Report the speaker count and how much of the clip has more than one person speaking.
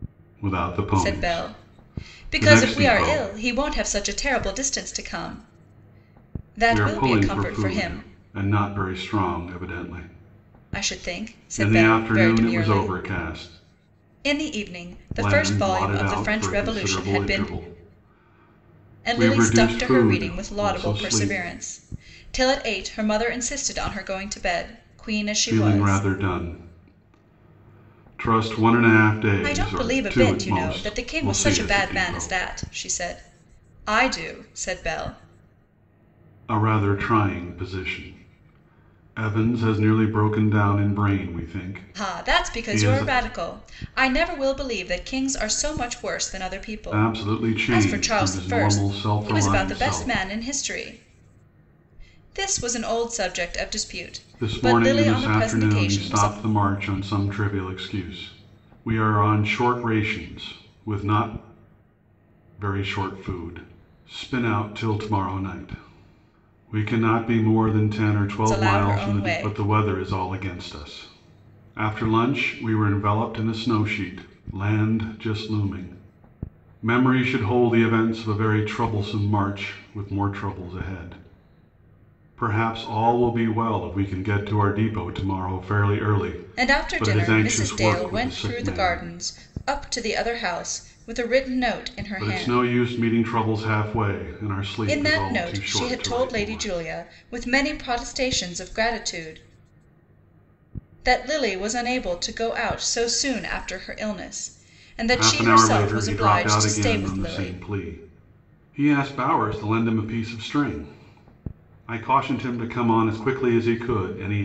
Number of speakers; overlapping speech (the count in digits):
2, about 26%